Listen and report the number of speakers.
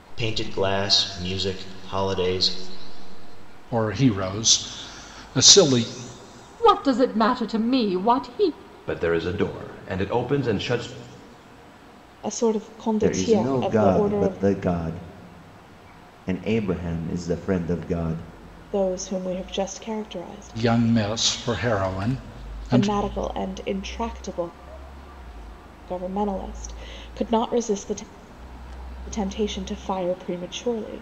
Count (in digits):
6